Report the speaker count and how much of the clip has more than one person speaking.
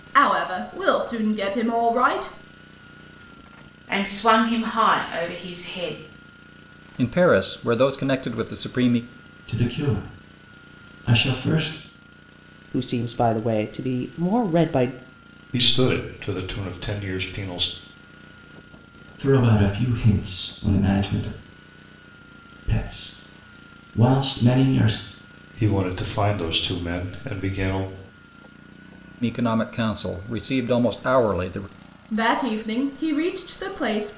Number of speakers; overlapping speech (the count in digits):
6, no overlap